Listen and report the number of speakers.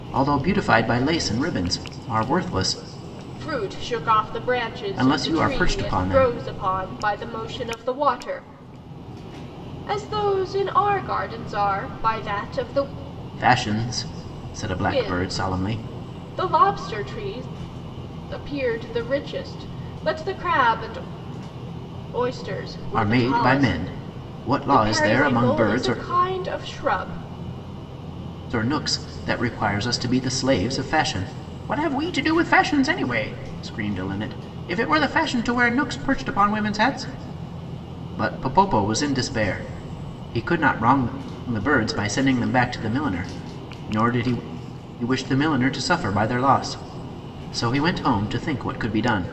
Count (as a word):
two